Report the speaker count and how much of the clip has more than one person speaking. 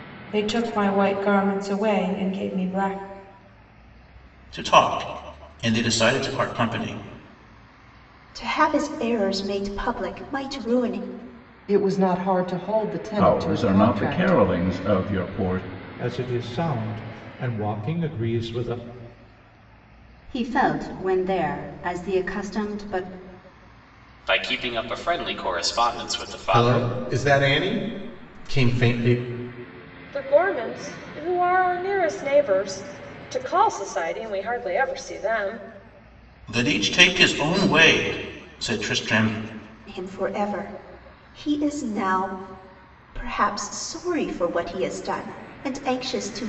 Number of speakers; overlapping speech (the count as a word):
ten, about 4%